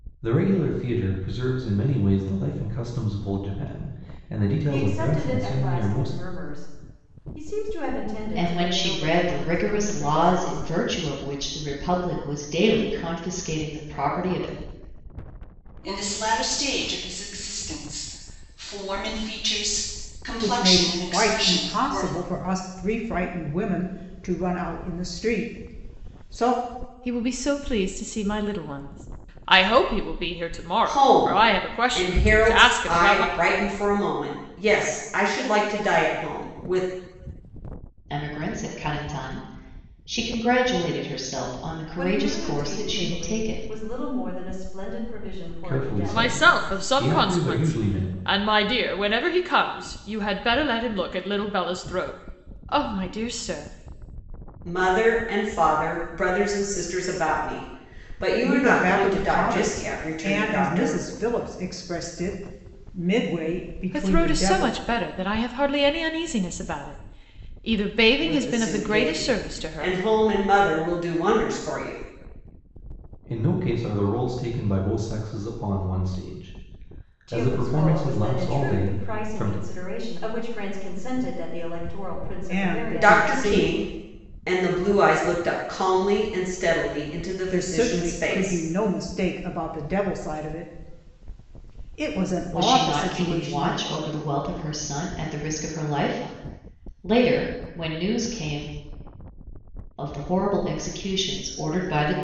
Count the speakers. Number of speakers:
7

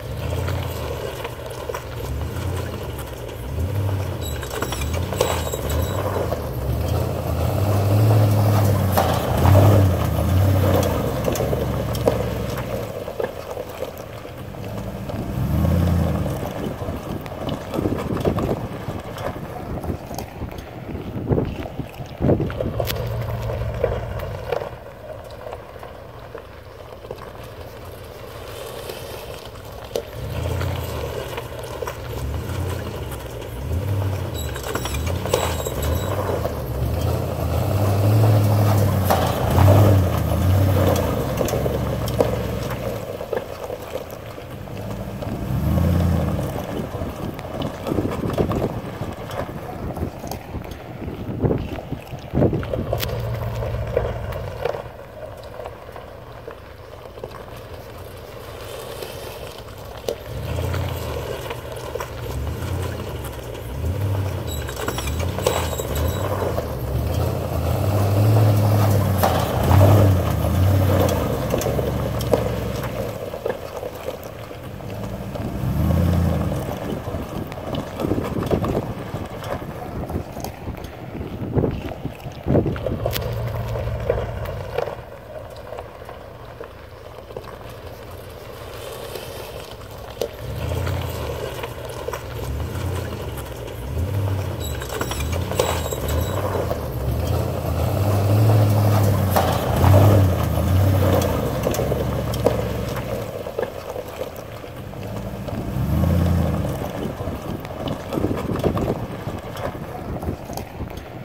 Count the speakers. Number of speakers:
0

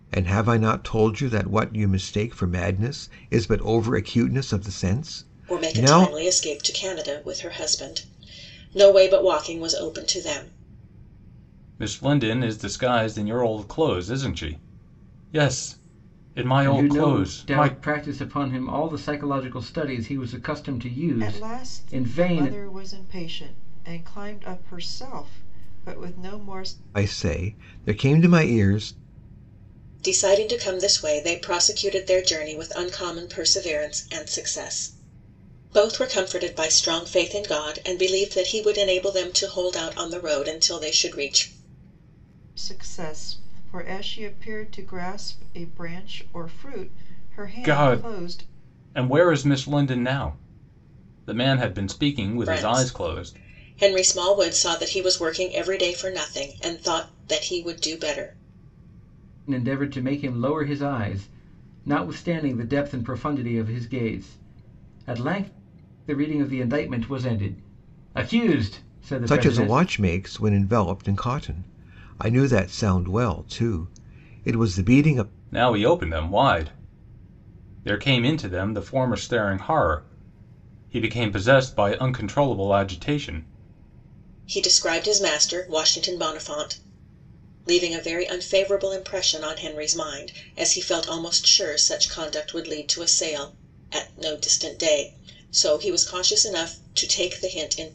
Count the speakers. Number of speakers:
5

